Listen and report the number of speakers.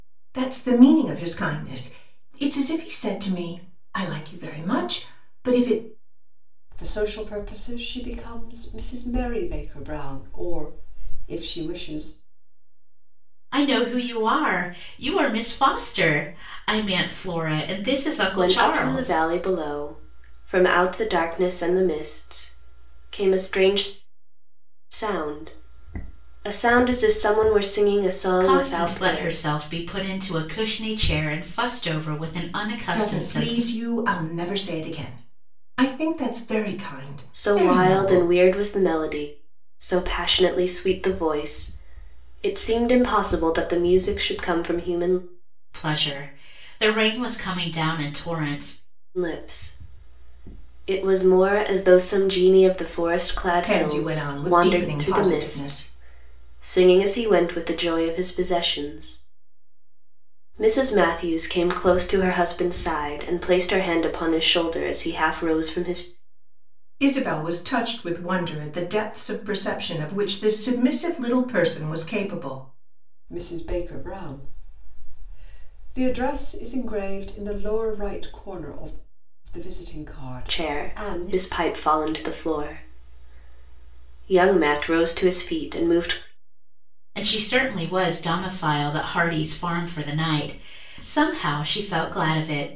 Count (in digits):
4